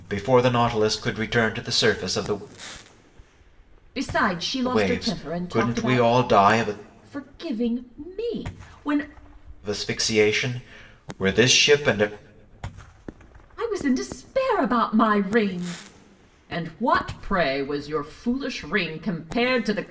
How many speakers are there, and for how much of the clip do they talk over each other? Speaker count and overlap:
2, about 7%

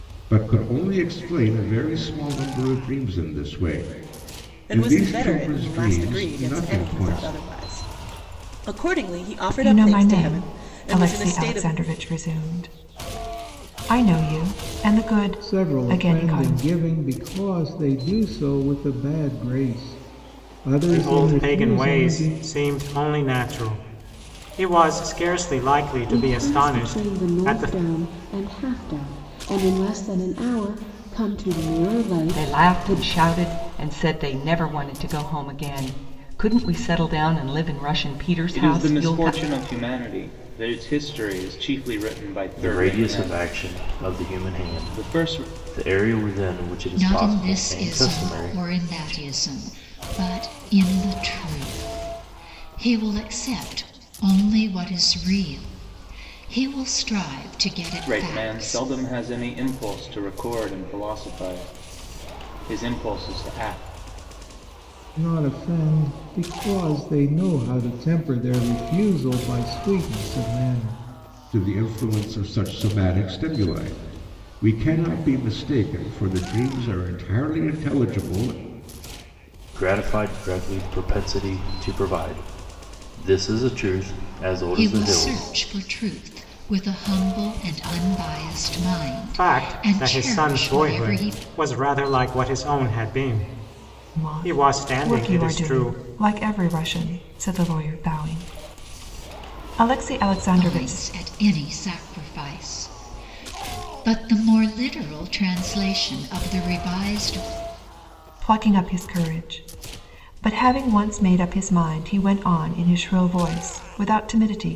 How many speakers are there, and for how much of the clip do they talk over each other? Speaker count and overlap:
10, about 19%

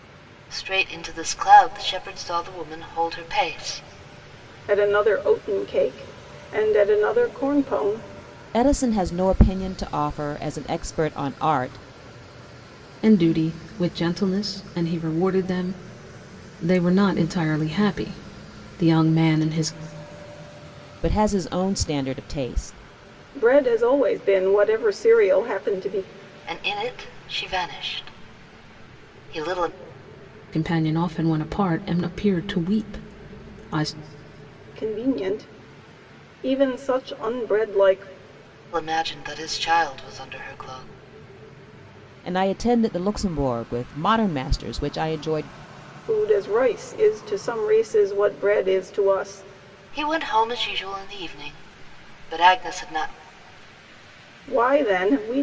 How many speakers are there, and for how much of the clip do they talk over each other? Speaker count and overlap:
4, no overlap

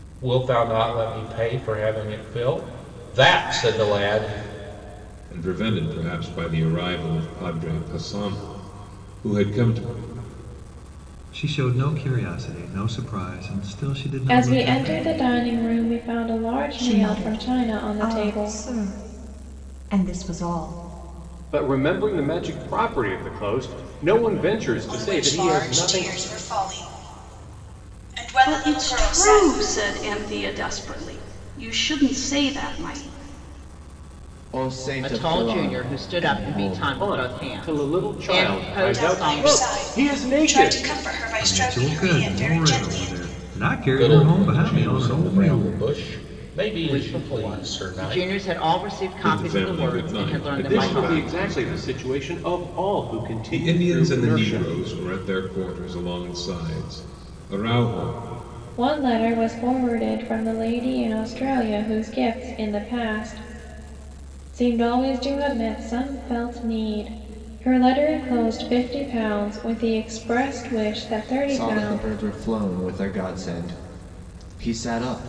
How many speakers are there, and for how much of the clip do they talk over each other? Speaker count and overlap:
10, about 28%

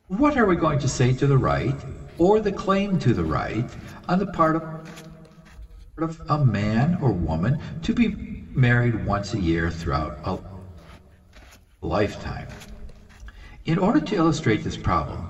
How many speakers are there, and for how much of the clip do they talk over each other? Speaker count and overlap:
1, no overlap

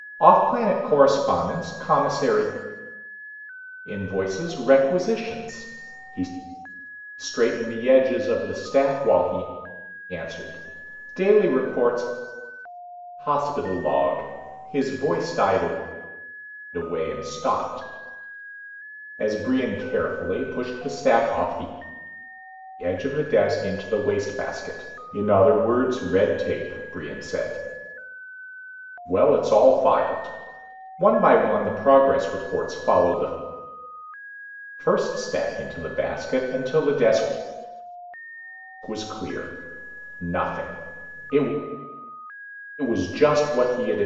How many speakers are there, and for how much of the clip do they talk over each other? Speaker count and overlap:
1, no overlap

